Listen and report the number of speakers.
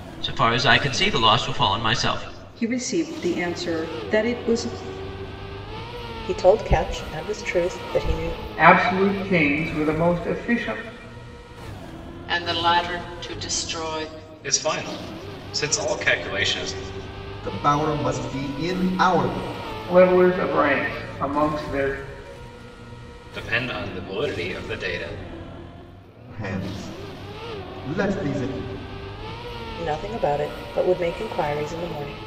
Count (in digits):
7